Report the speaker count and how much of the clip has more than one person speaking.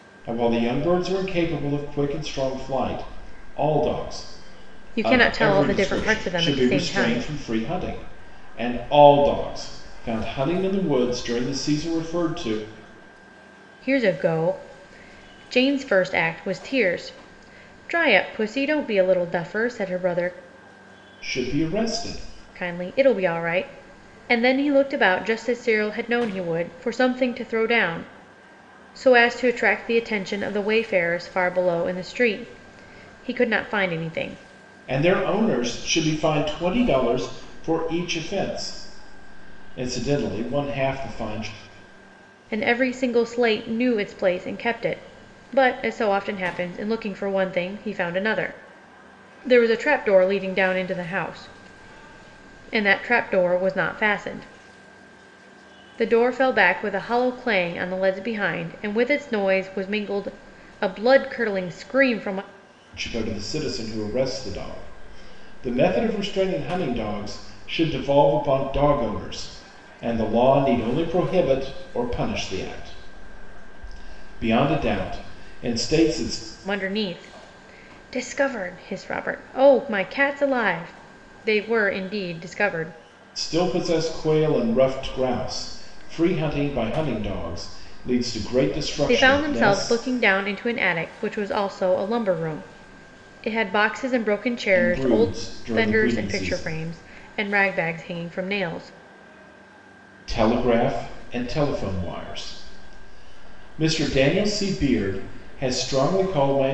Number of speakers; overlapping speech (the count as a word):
two, about 5%